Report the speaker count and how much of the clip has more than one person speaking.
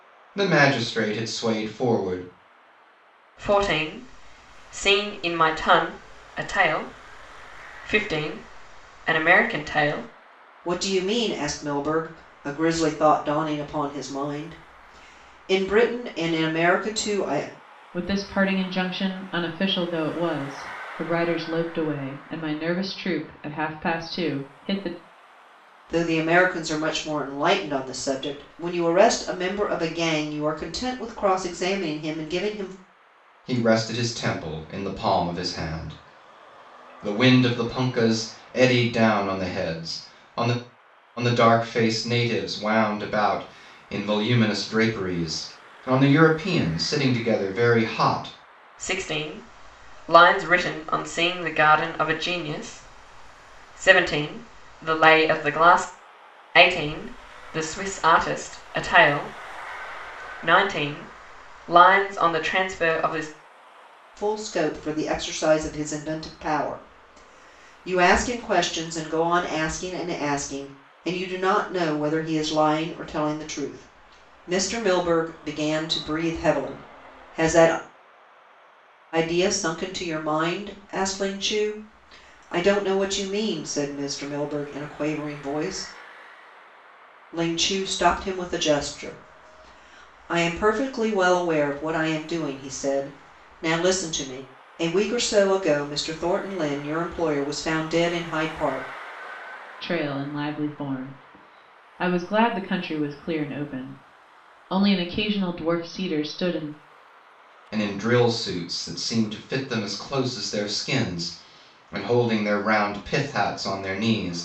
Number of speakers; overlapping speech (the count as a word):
four, no overlap